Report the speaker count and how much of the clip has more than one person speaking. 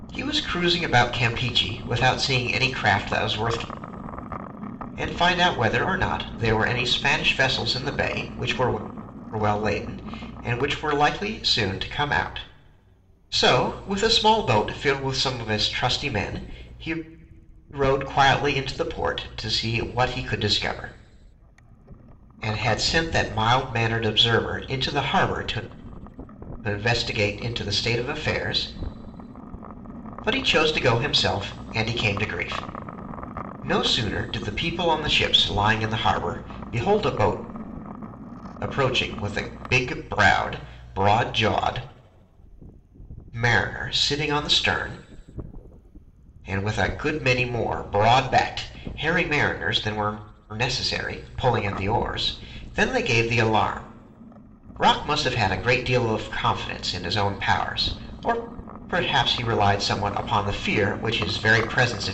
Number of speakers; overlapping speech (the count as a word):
one, no overlap